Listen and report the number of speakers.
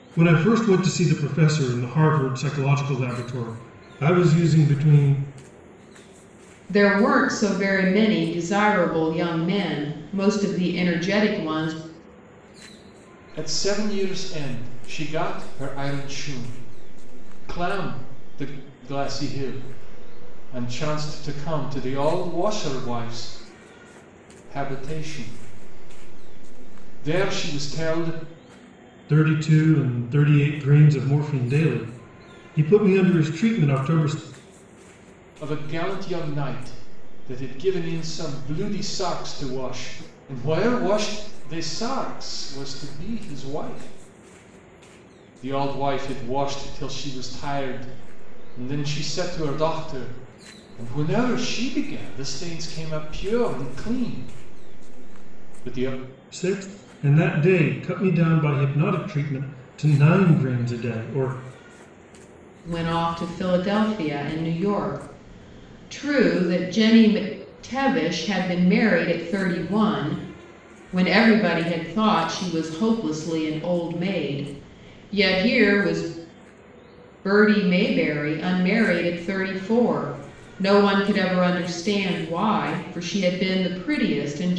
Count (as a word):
three